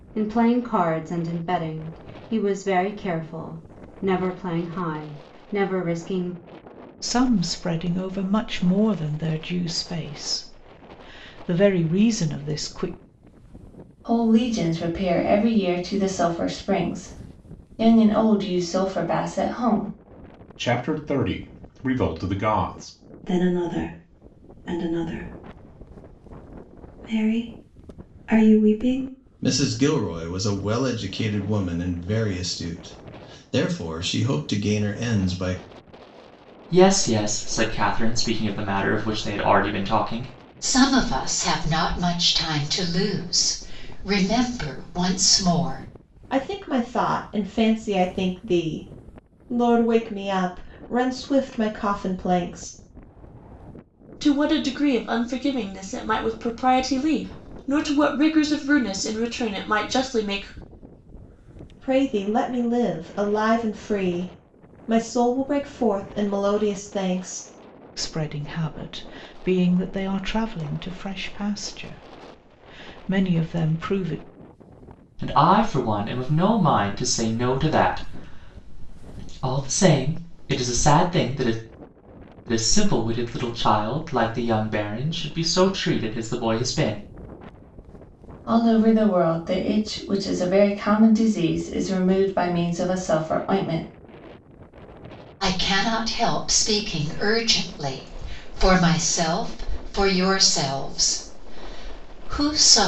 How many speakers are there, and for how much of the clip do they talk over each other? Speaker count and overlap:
ten, no overlap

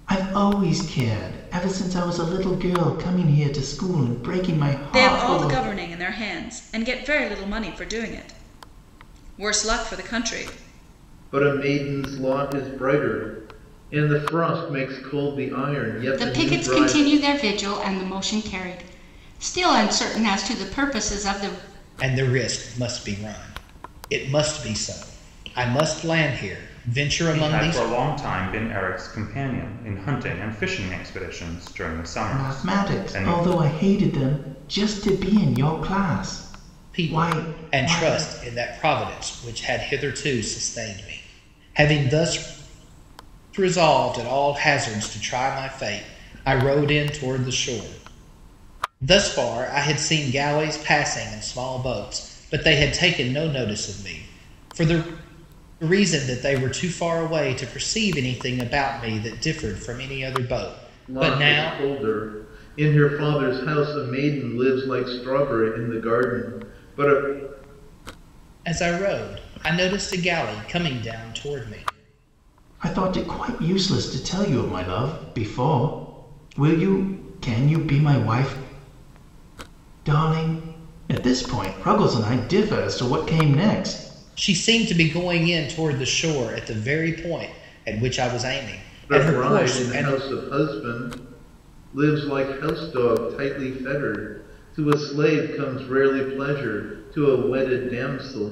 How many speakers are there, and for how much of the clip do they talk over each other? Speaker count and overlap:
six, about 7%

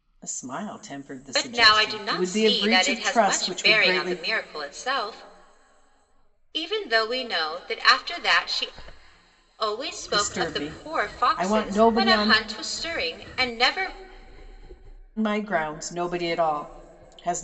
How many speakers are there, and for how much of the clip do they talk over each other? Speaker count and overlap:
two, about 30%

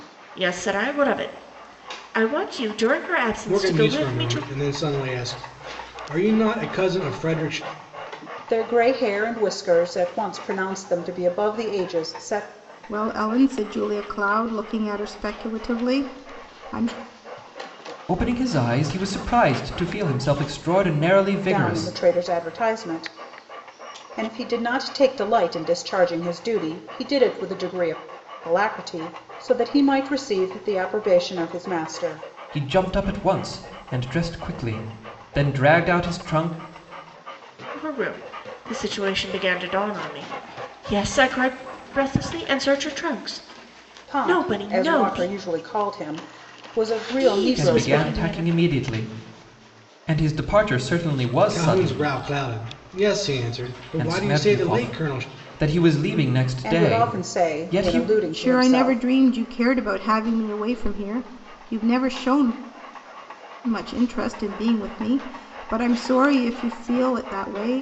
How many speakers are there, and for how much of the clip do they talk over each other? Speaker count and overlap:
five, about 12%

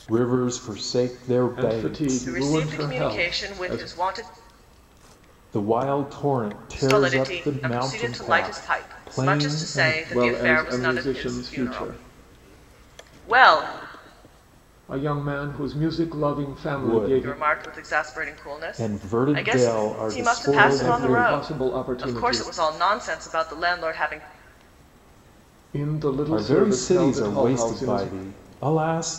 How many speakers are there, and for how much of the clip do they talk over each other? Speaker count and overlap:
three, about 49%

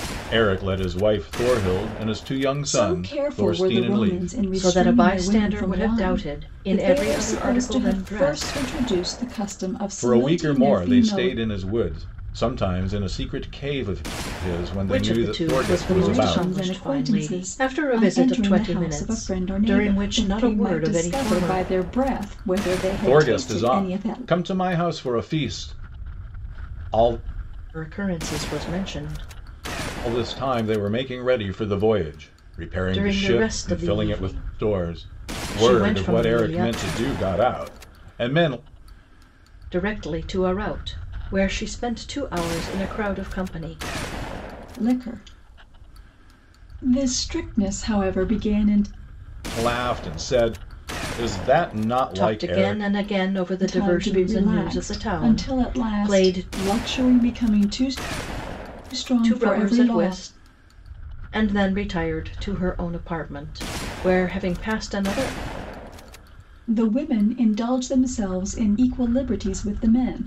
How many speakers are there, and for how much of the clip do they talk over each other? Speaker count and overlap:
three, about 34%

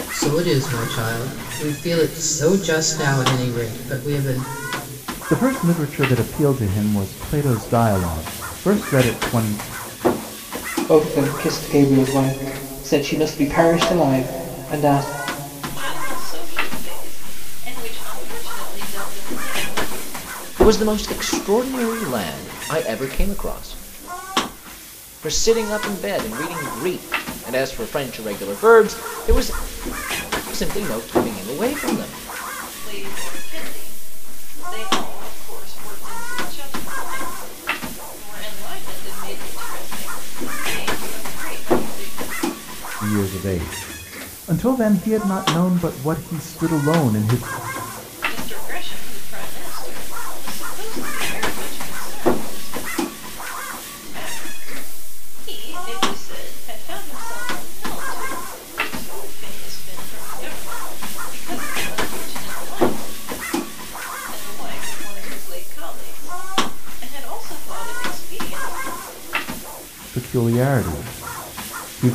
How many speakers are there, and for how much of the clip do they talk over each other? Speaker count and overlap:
five, no overlap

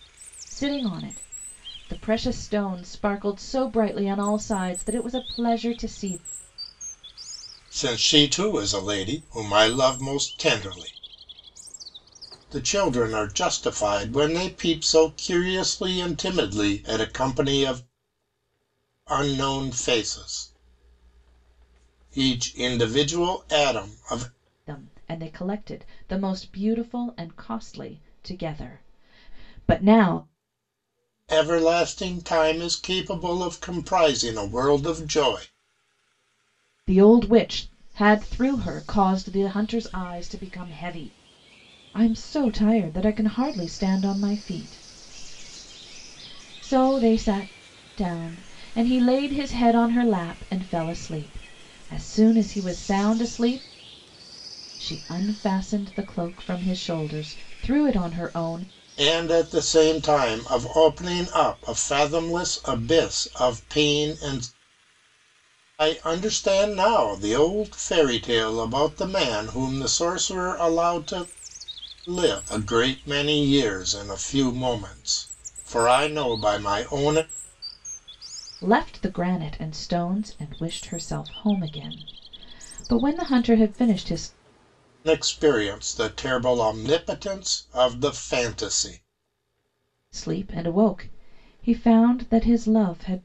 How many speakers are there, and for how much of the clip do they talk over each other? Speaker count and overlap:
two, no overlap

